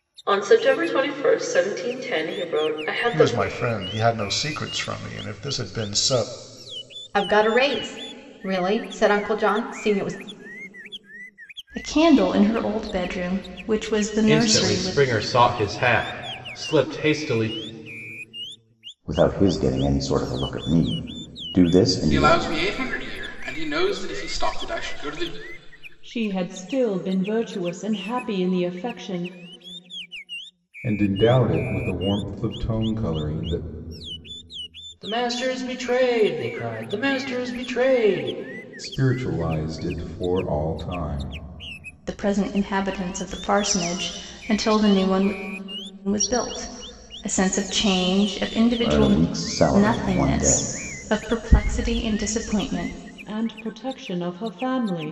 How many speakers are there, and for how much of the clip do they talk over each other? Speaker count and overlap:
ten, about 5%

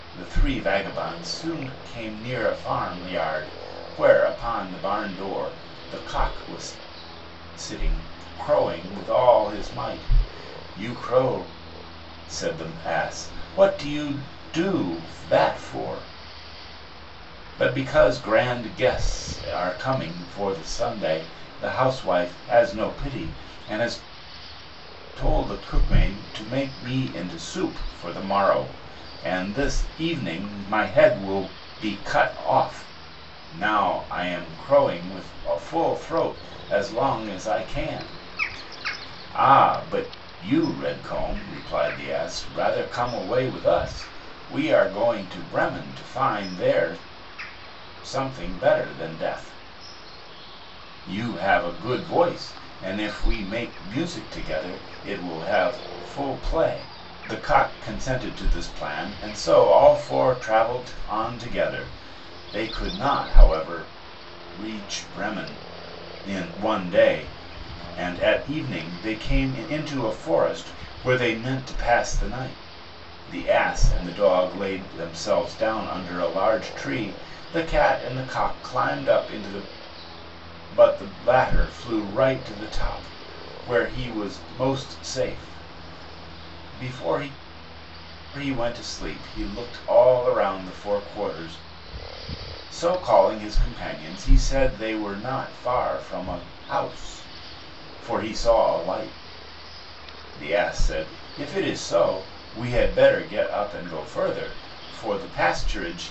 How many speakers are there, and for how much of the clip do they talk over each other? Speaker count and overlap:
one, no overlap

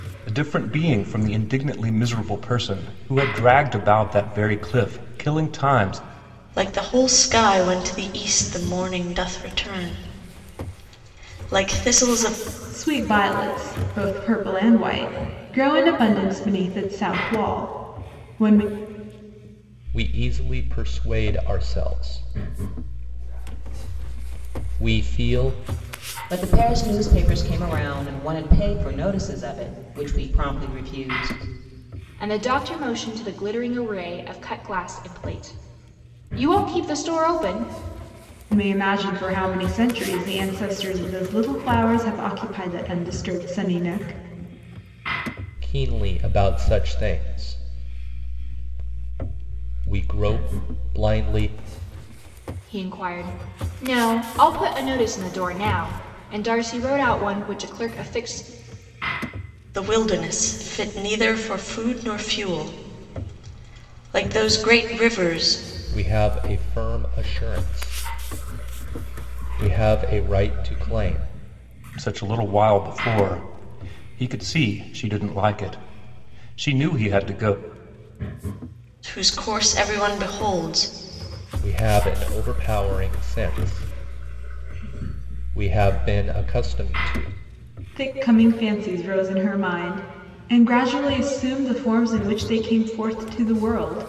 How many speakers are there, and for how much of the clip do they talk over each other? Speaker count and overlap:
six, no overlap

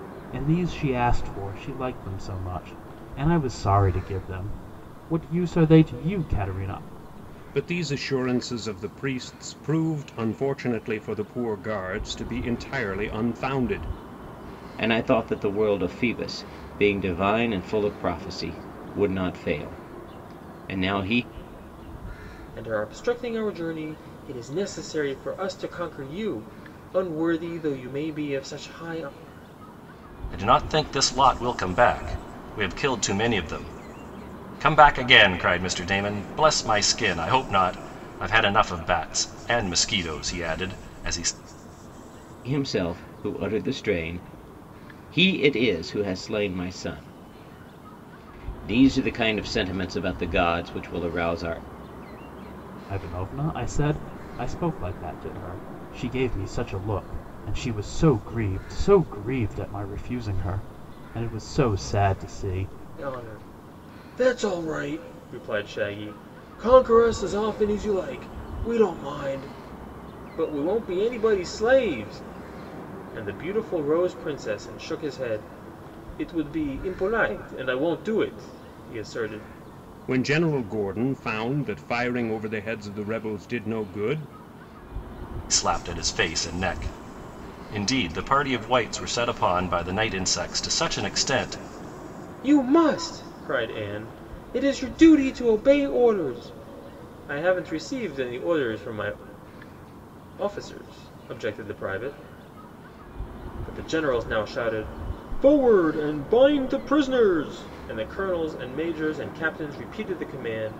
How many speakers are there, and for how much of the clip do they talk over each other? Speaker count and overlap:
five, no overlap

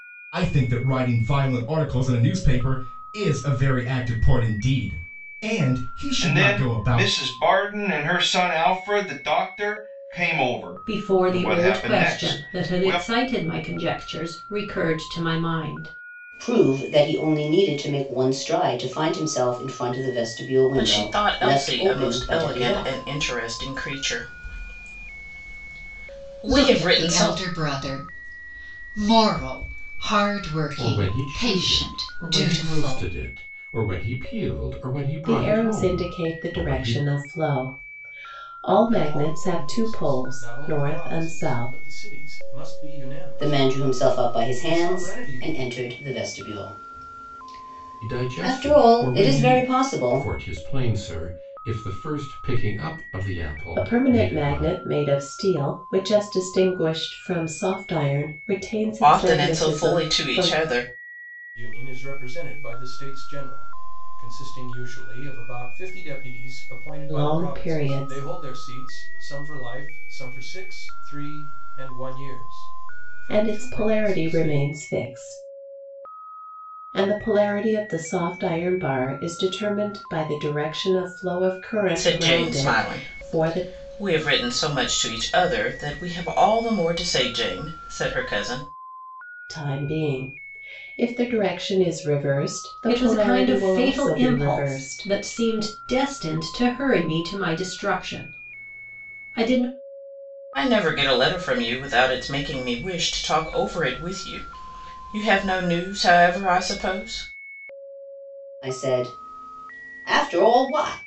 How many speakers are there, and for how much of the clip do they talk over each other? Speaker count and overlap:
nine, about 25%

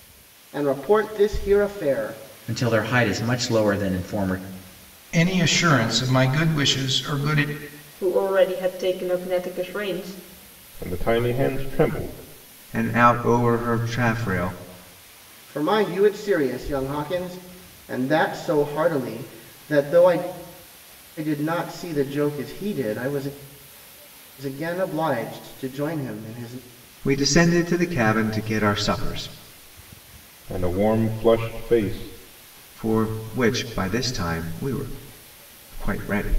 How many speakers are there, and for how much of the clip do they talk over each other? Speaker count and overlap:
six, no overlap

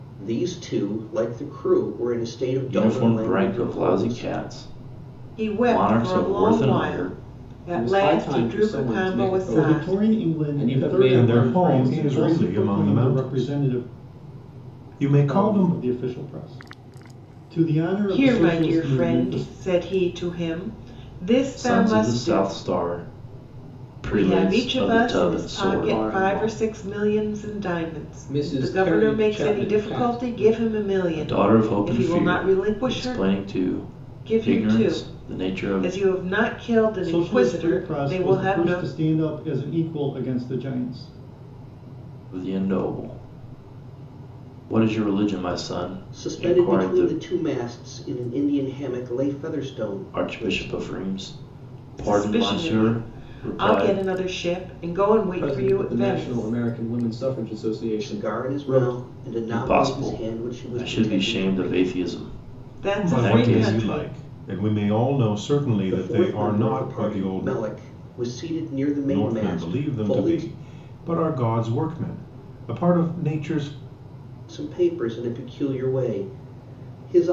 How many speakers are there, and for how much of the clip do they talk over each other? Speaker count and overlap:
six, about 48%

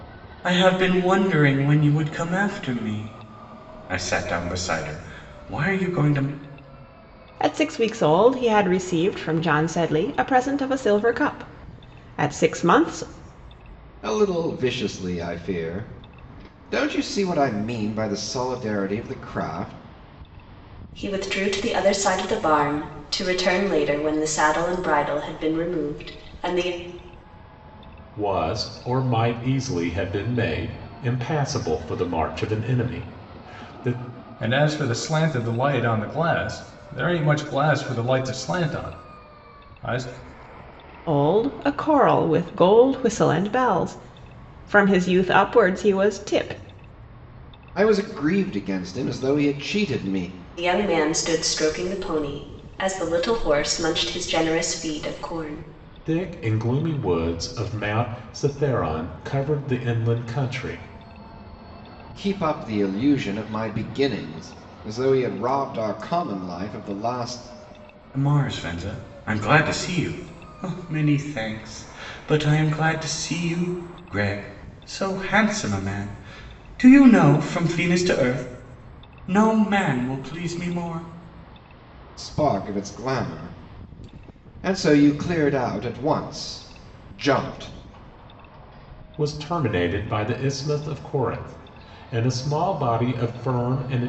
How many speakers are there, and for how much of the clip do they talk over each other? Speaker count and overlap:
six, no overlap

